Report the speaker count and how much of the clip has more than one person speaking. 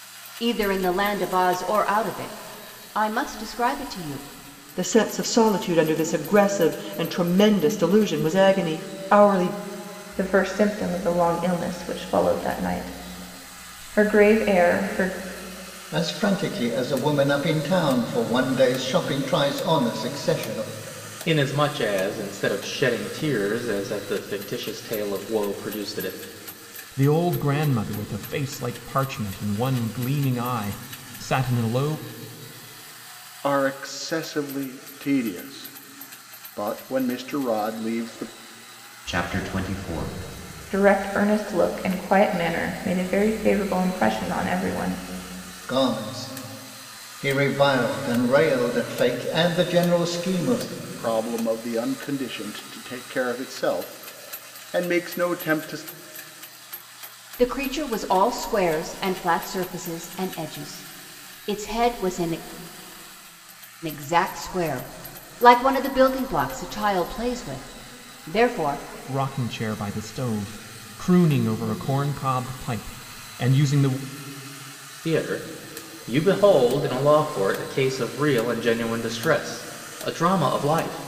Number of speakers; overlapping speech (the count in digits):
8, no overlap